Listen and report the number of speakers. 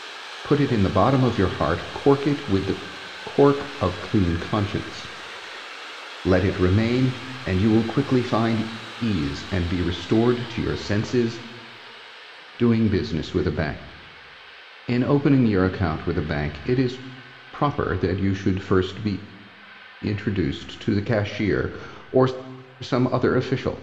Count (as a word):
one